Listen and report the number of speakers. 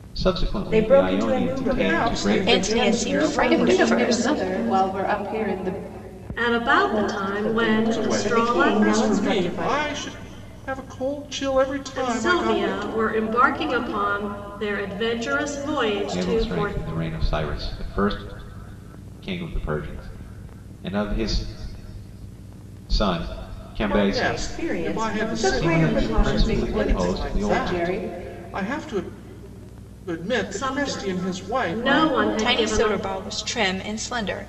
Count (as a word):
seven